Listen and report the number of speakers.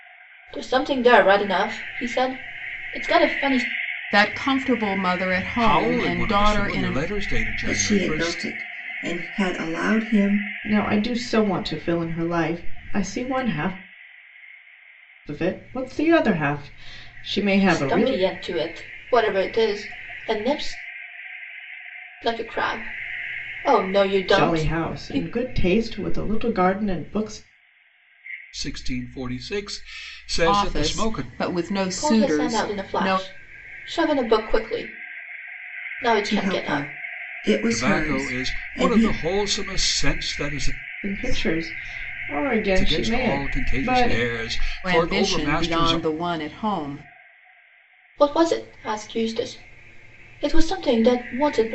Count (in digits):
5